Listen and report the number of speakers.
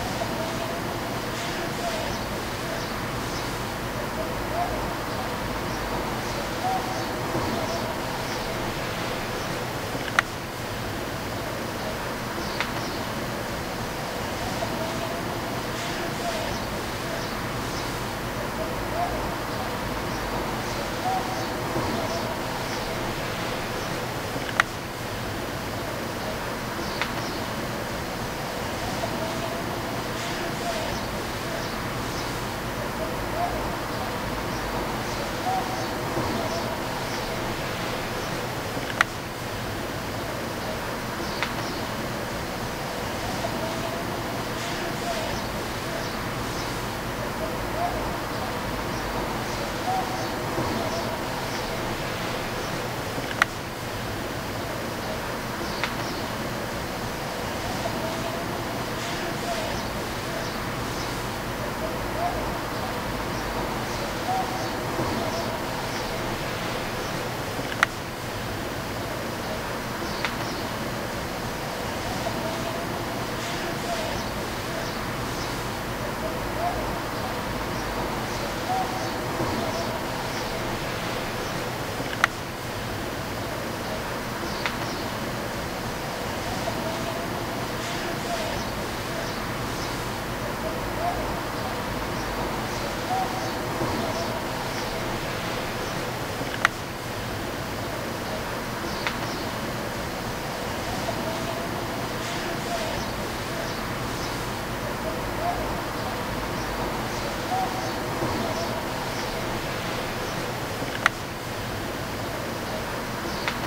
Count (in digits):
0